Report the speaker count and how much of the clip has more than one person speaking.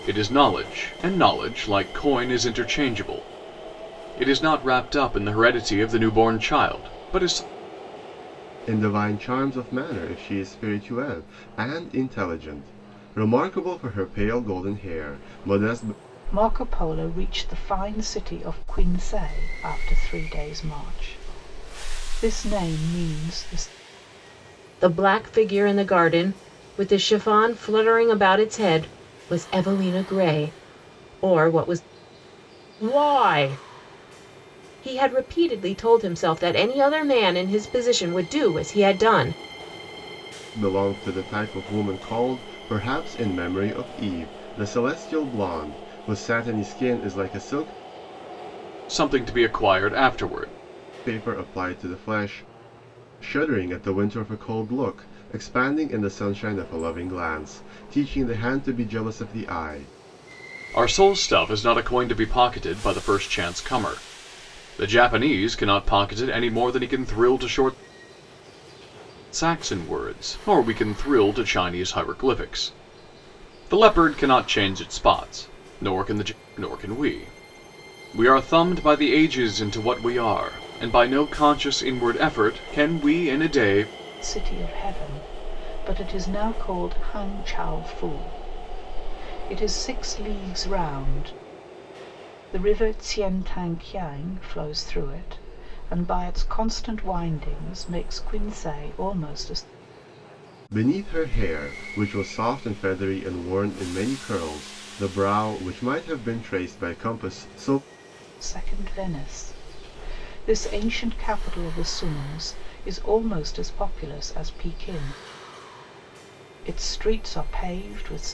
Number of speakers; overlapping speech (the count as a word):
four, no overlap